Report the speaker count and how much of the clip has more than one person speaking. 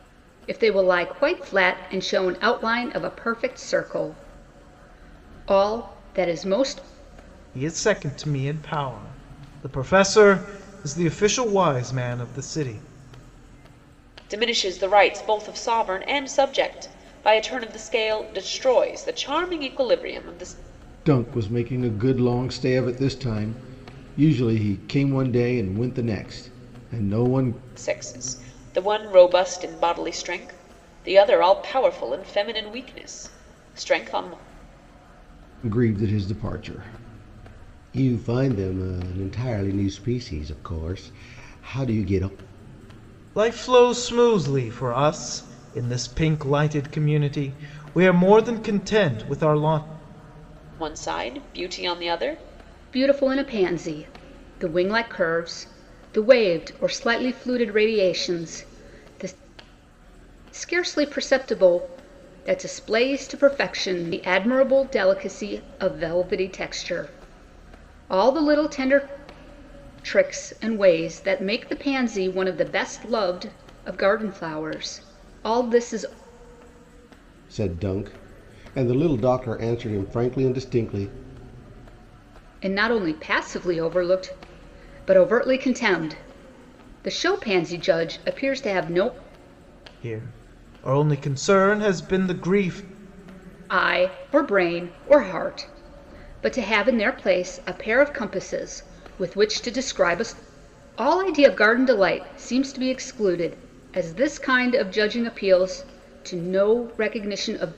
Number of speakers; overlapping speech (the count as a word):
four, no overlap